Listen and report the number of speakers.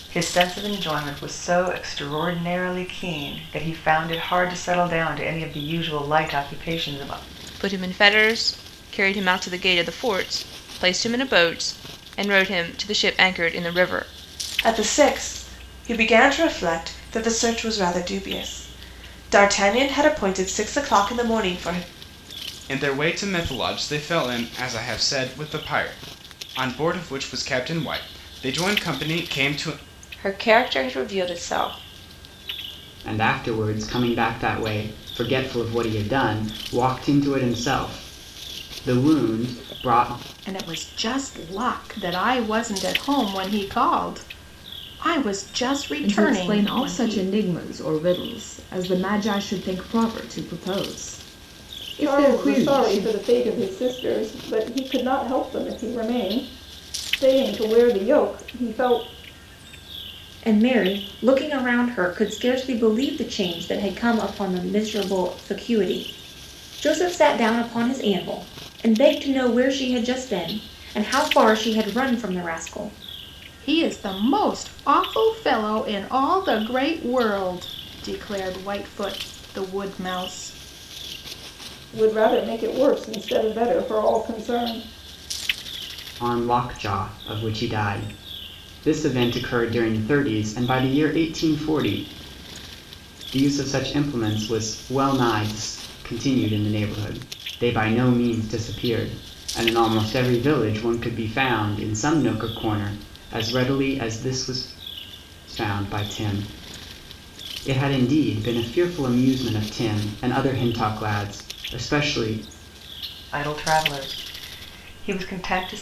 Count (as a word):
ten